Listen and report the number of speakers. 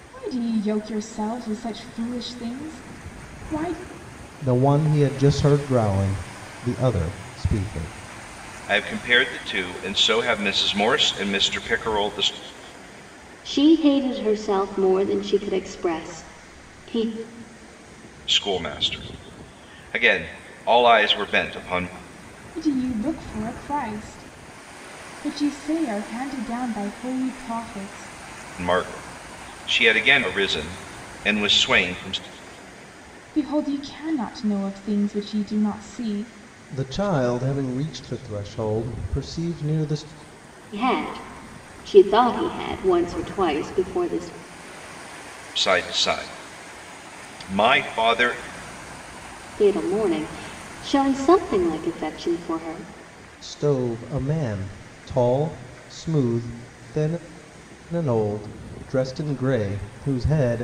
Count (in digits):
4